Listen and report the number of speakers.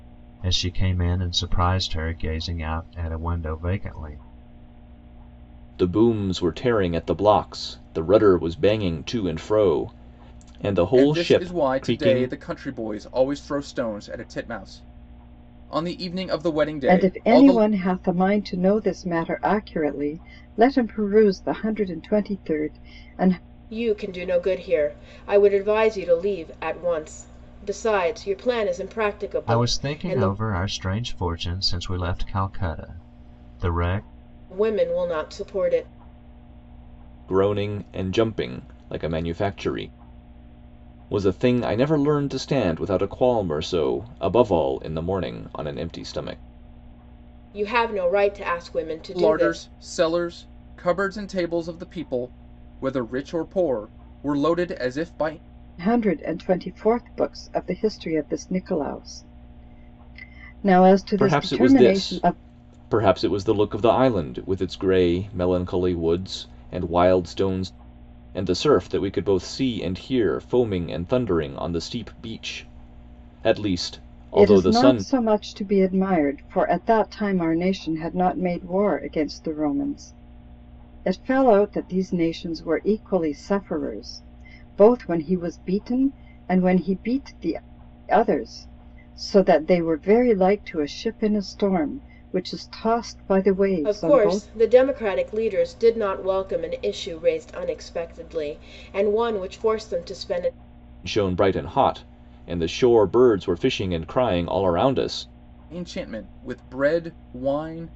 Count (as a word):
five